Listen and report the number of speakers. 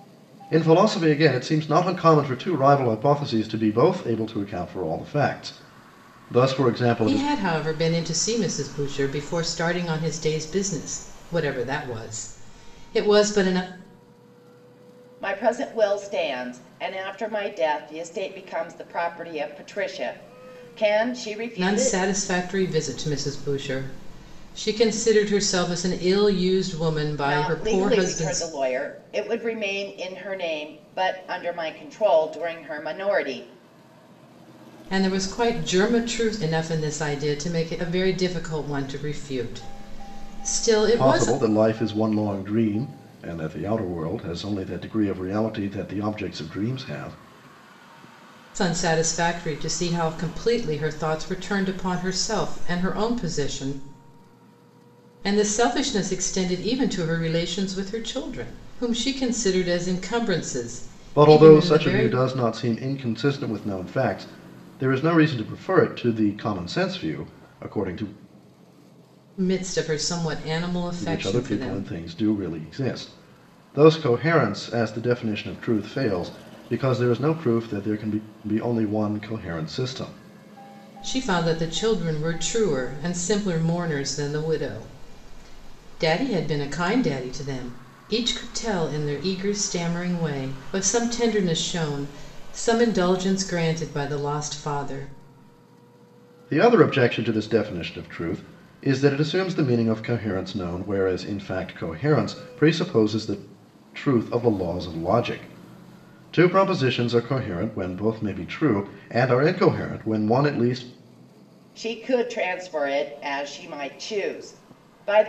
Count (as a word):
three